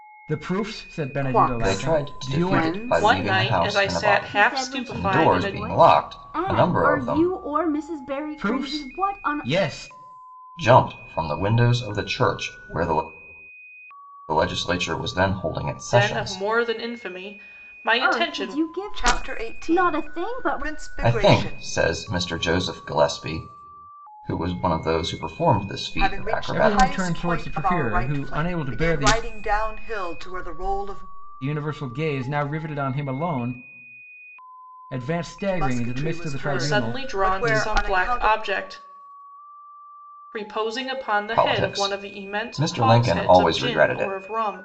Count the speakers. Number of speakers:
5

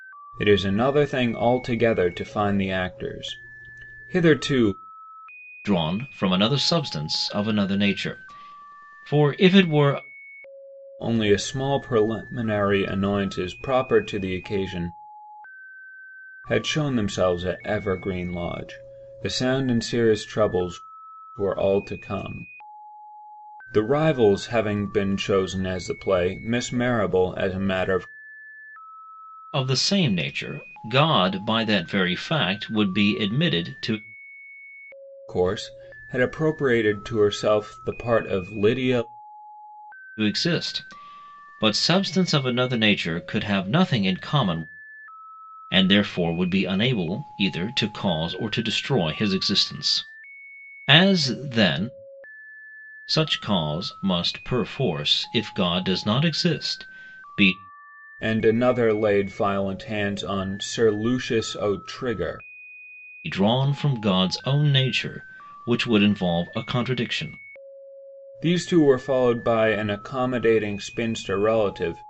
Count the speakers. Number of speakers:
2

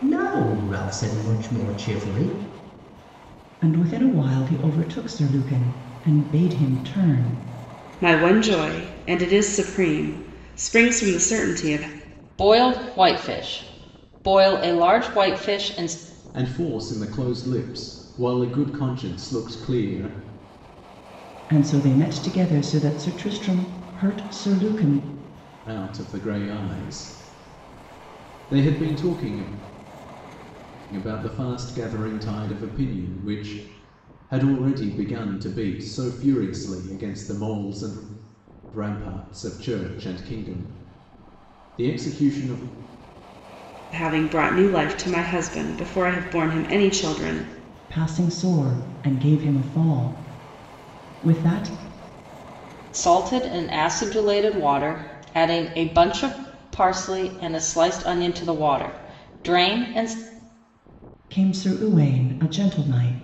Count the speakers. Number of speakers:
5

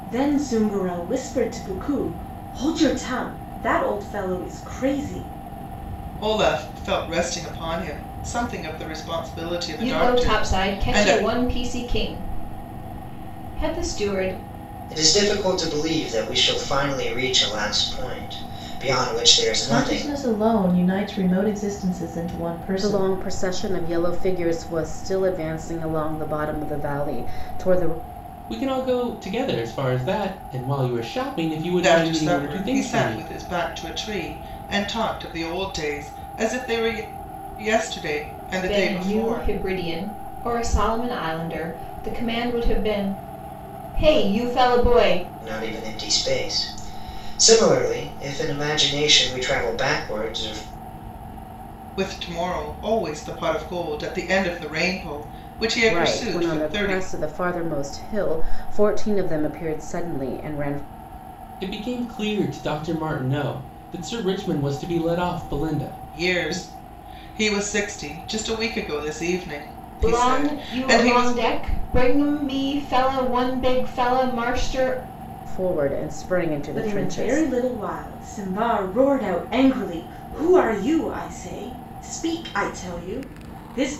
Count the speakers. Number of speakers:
7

